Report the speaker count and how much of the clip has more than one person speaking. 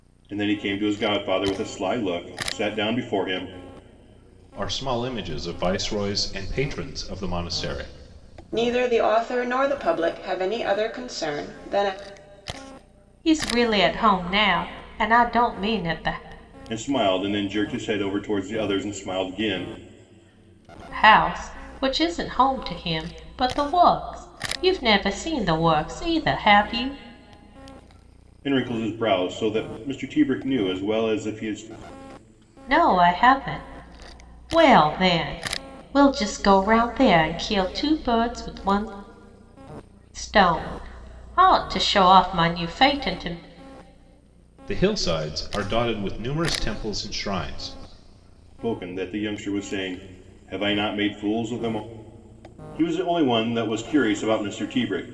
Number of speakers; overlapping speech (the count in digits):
4, no overlap